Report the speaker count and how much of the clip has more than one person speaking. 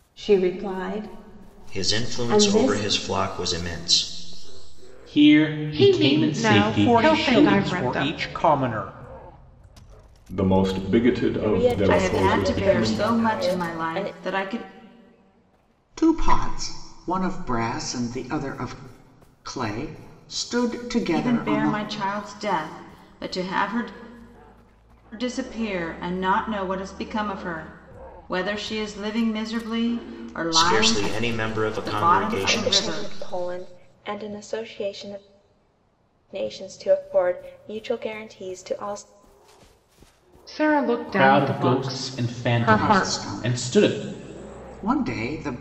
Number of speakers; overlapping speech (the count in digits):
9, about 27%